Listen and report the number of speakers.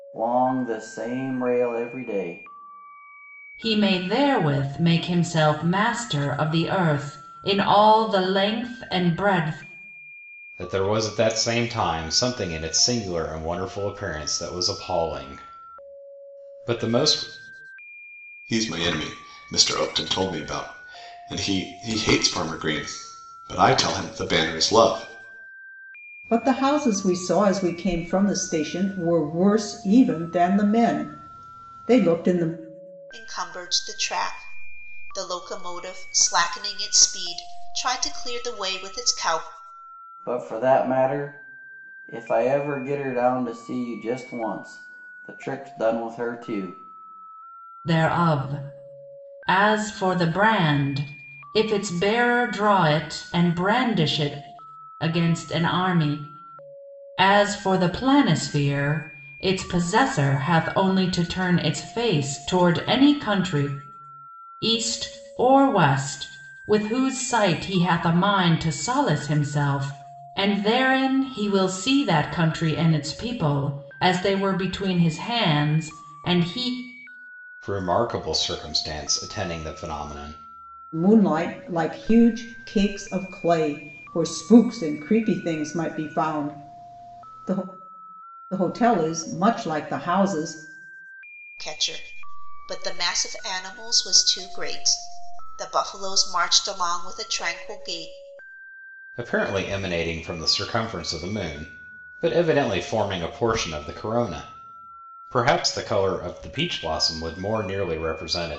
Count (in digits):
6